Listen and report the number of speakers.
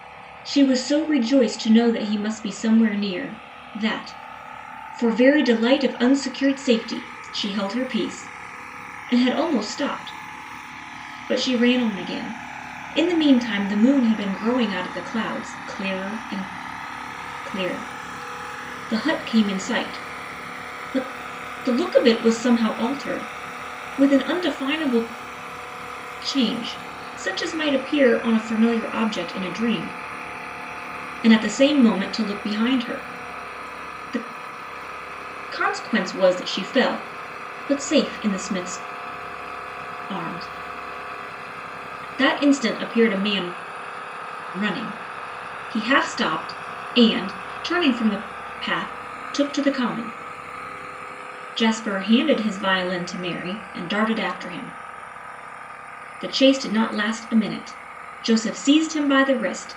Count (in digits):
1